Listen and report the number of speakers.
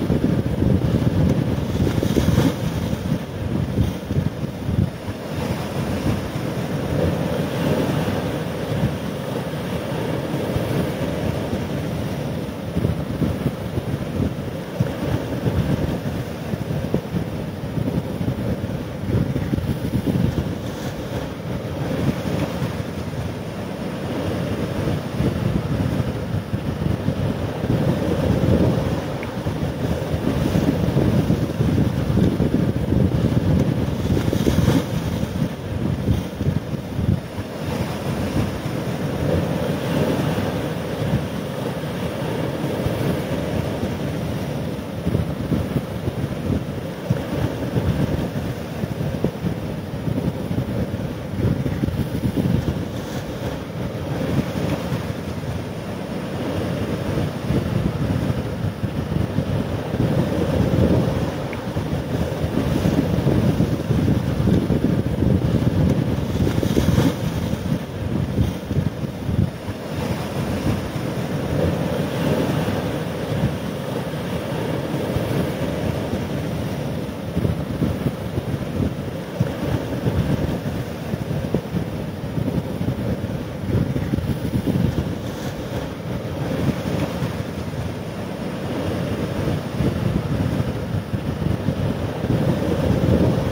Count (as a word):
zero